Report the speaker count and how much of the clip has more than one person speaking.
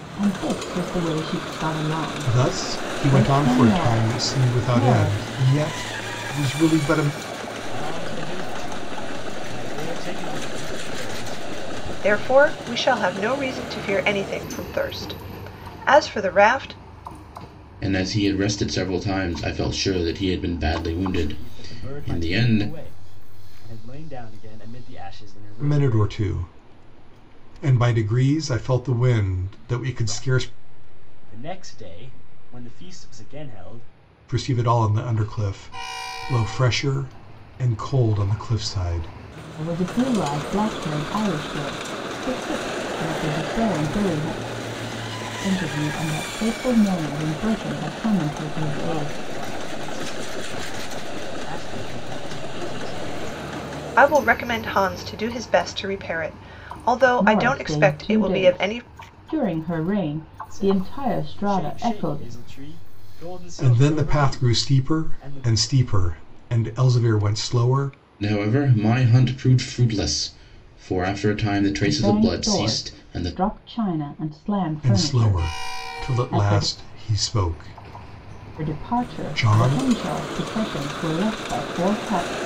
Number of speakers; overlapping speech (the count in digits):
5, about 21%